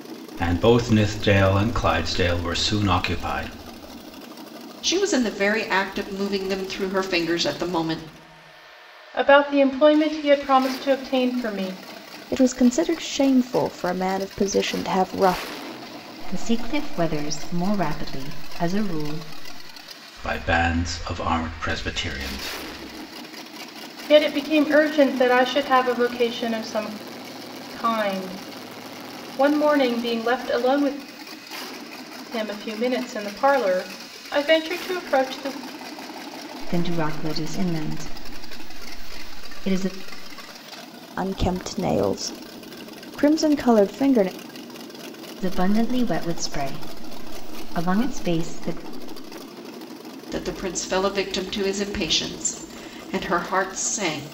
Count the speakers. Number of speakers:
5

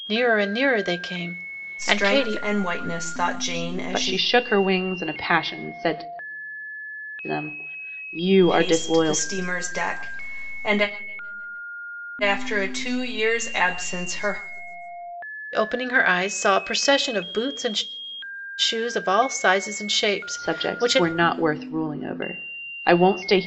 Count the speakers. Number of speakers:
3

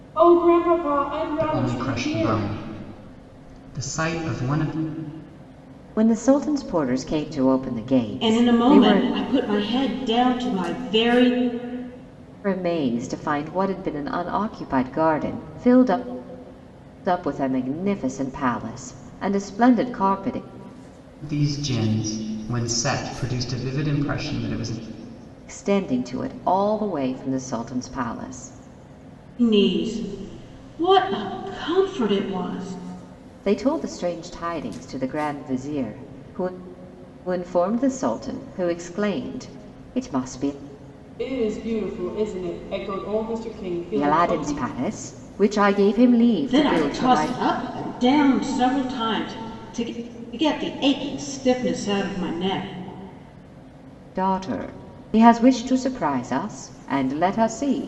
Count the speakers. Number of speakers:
4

